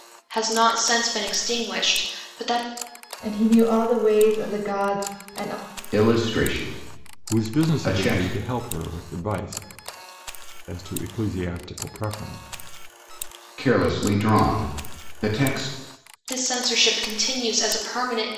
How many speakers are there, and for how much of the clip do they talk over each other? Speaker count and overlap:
four, about 6%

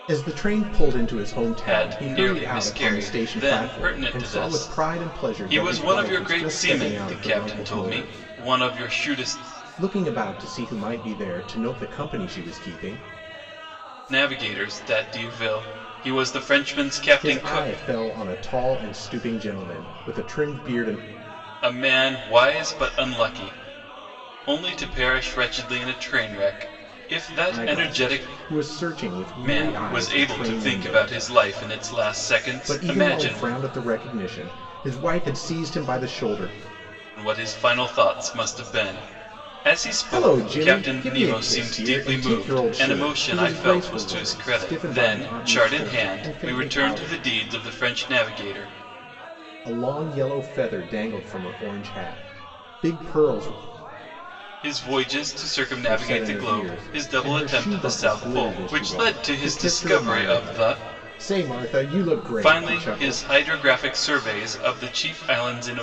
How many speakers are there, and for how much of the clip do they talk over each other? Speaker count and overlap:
two, about 35%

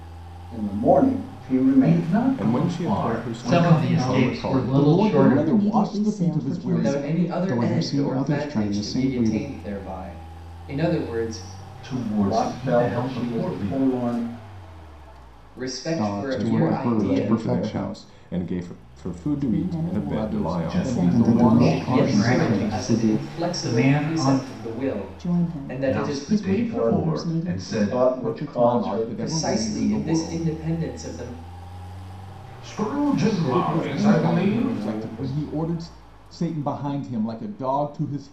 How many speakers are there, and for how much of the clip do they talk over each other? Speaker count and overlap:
eight, about 63%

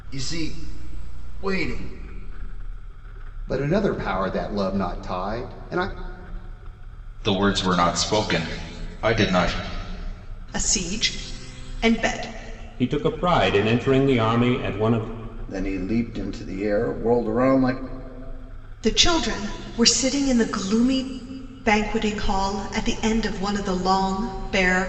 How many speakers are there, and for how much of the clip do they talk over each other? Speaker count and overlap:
six, no overlap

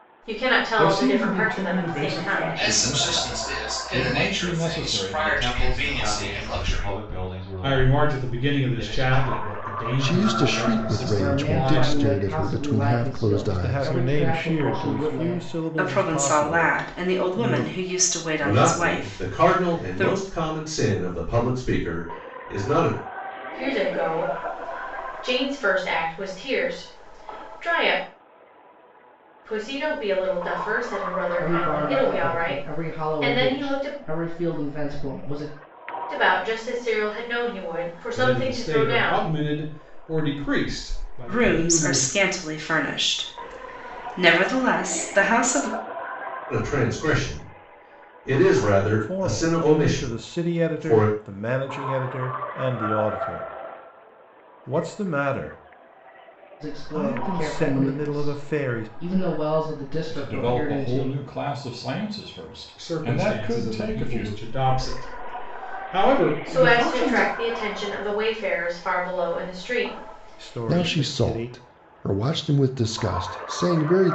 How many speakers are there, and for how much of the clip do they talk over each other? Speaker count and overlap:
ten, about 42%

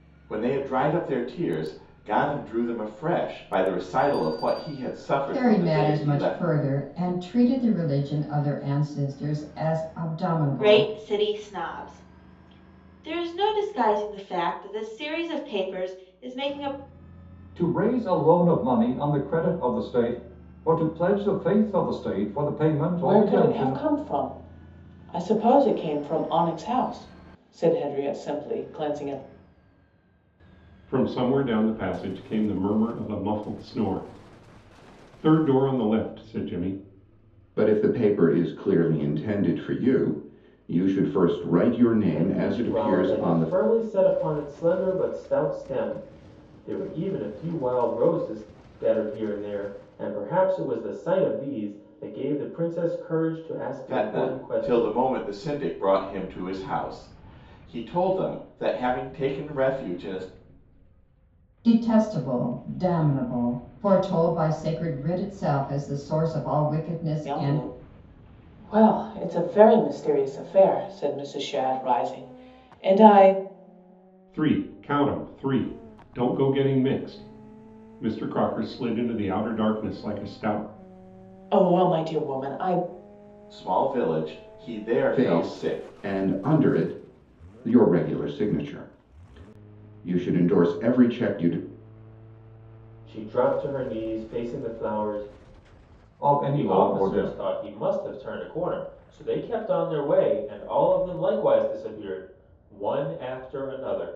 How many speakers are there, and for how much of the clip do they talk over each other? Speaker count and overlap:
eight, about 7%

